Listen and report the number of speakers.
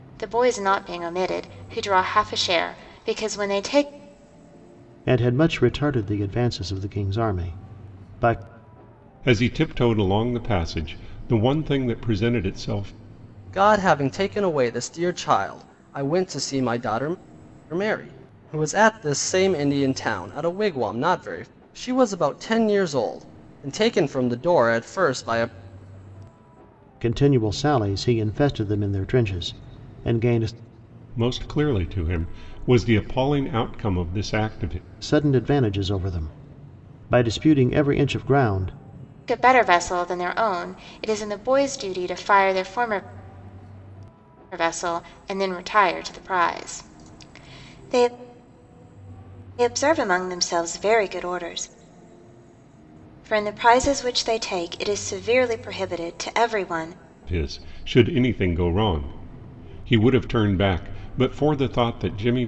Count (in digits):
4